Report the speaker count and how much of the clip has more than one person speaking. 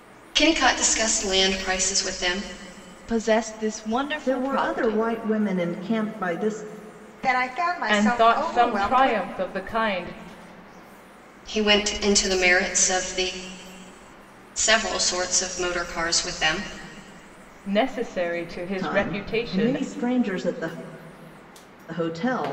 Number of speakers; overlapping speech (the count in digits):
5, about 15%